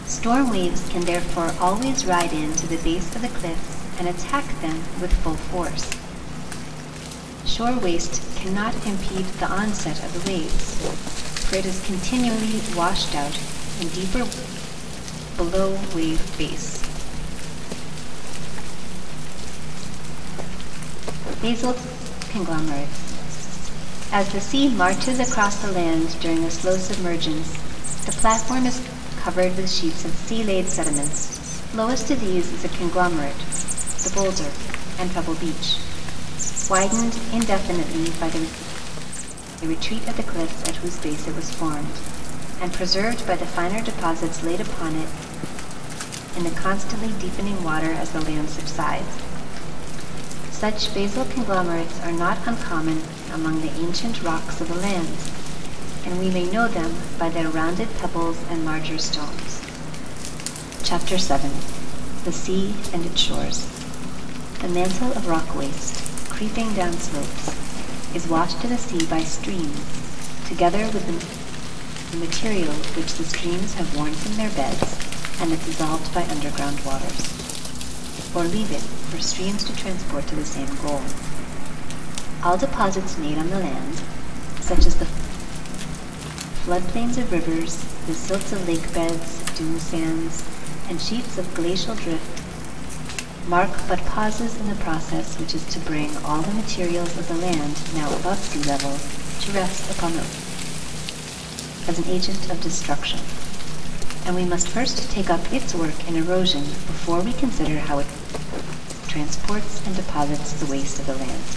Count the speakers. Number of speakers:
1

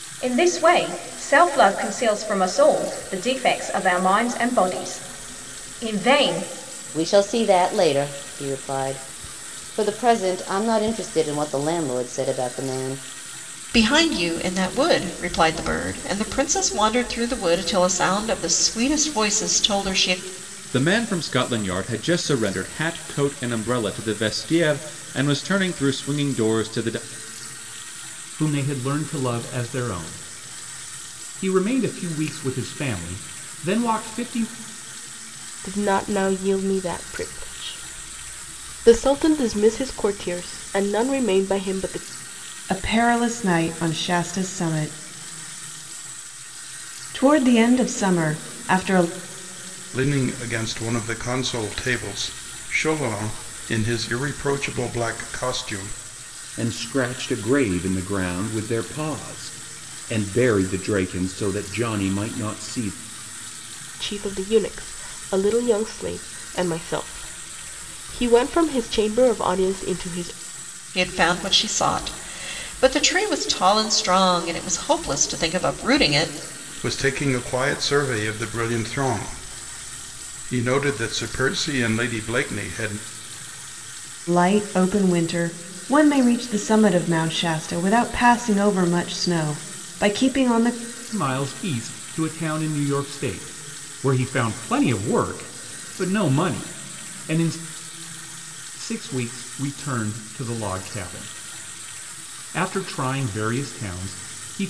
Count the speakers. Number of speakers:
9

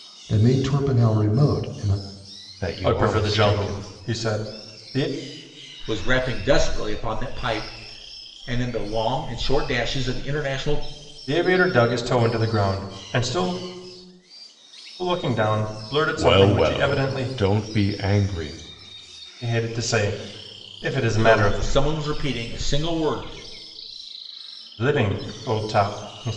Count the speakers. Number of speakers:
4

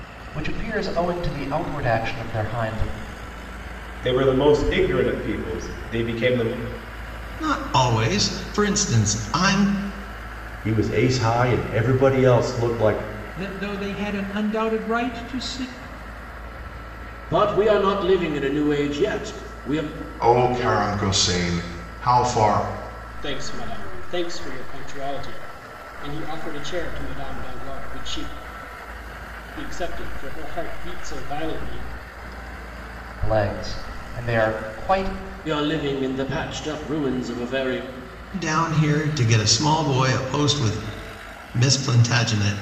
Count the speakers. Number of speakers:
8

